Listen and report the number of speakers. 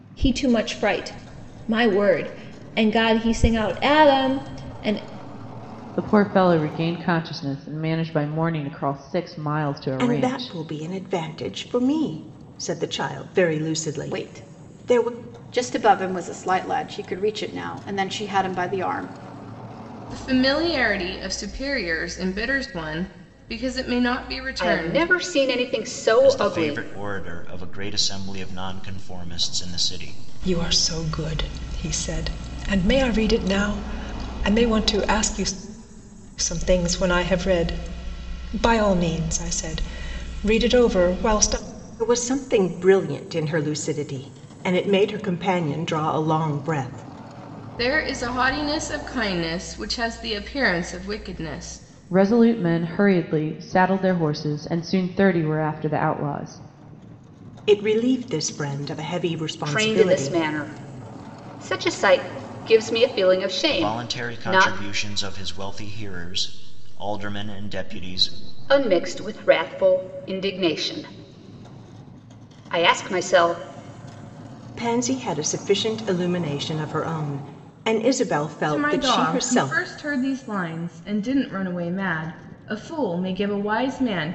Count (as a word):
eight